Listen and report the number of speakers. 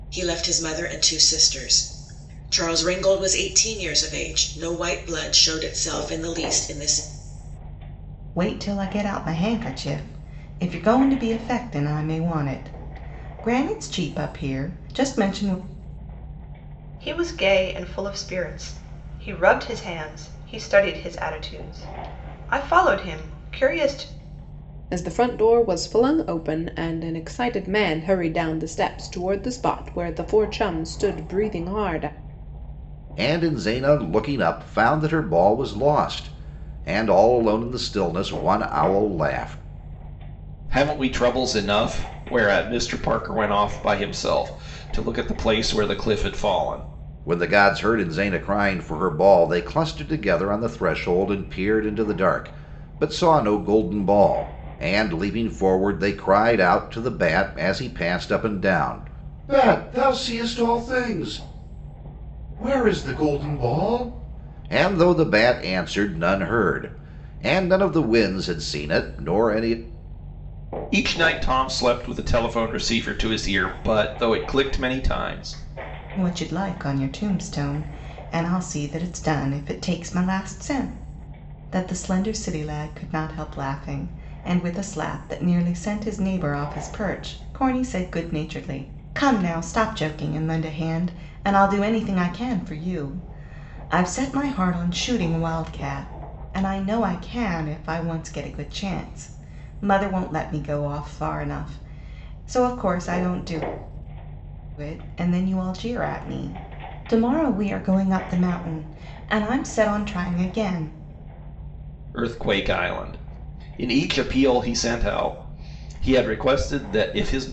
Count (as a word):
six